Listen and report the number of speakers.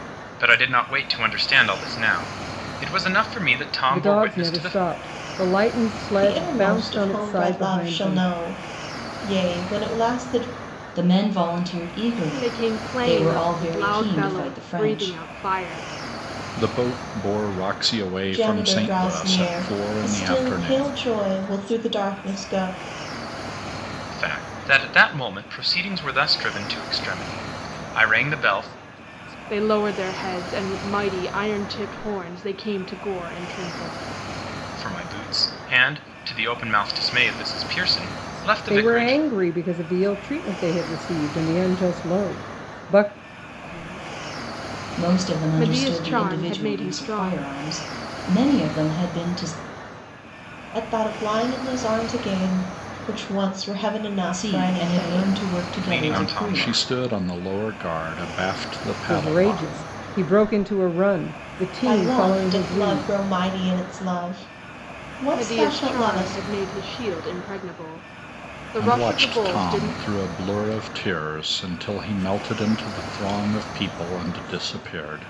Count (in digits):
6